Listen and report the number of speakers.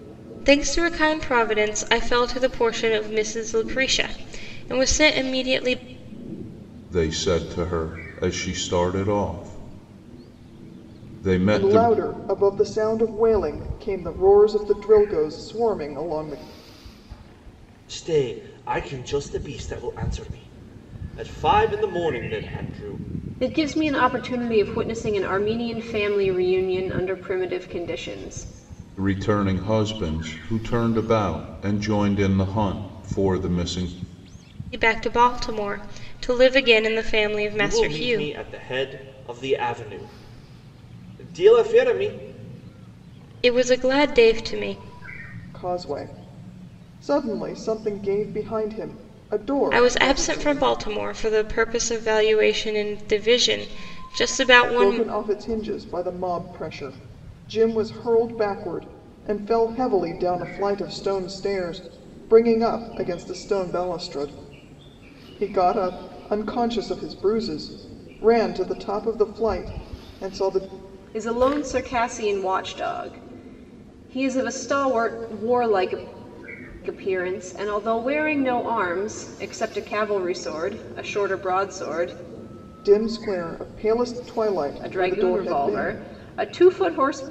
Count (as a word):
five